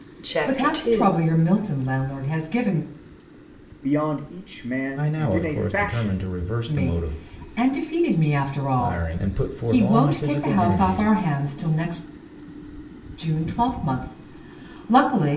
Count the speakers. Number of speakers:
4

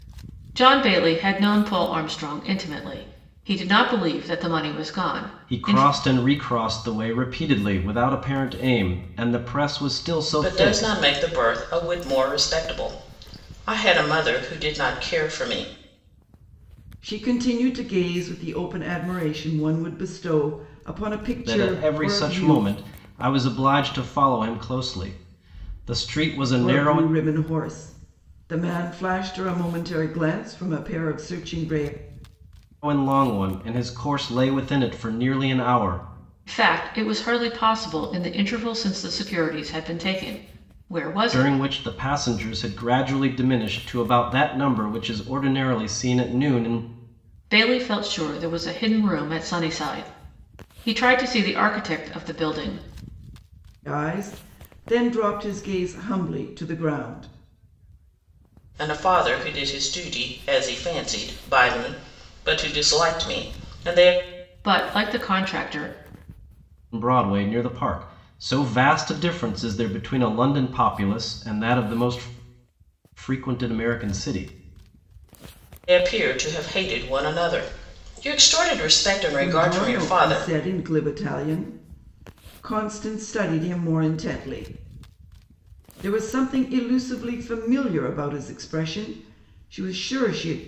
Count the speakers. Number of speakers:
4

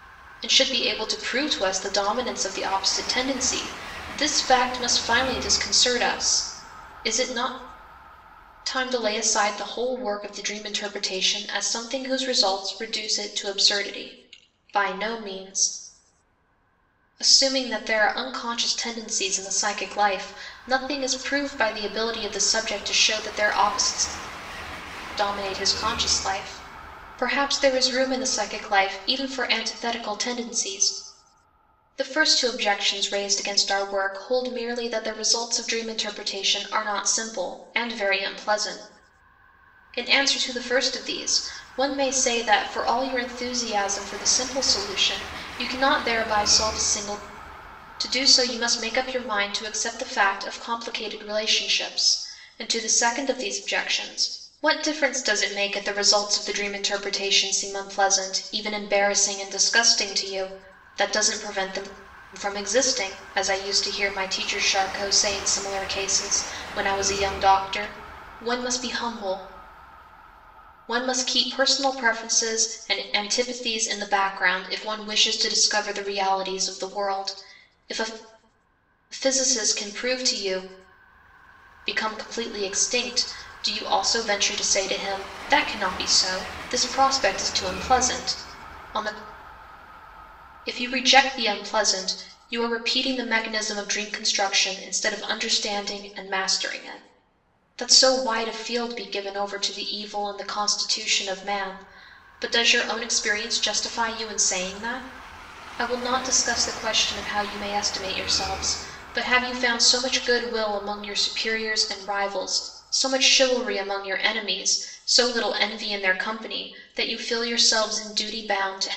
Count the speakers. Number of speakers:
1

